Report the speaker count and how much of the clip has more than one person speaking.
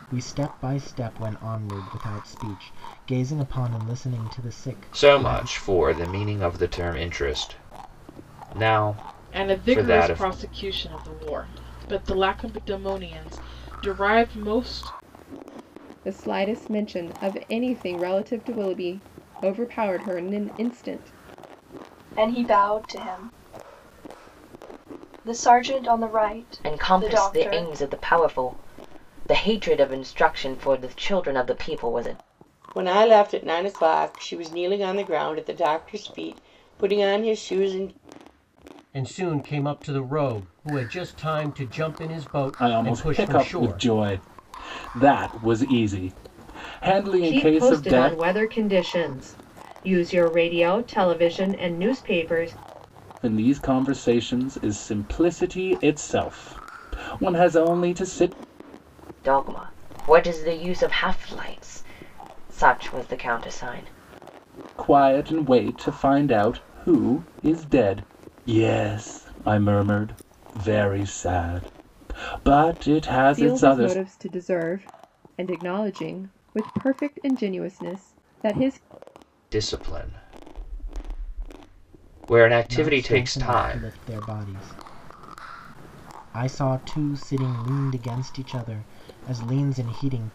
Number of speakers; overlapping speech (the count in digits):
10, about 8%